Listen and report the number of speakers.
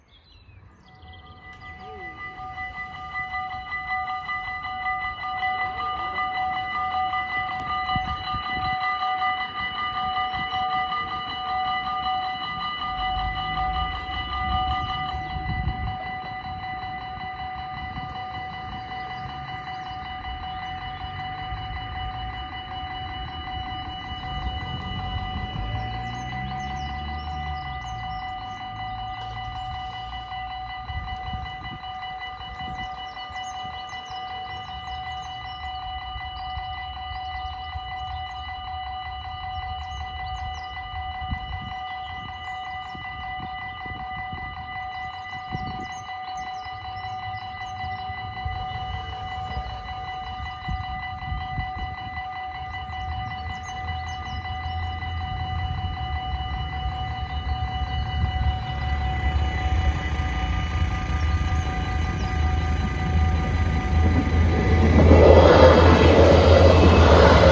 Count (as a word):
zero